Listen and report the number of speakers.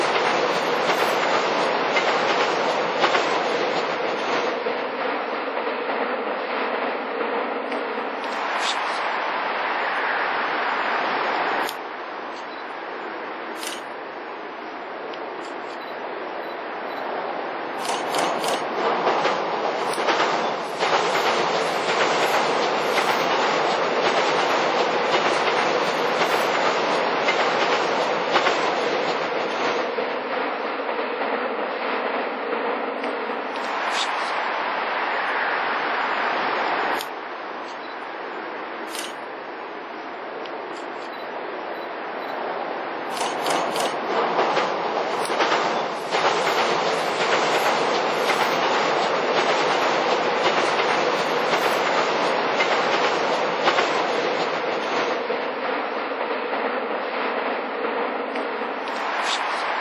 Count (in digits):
0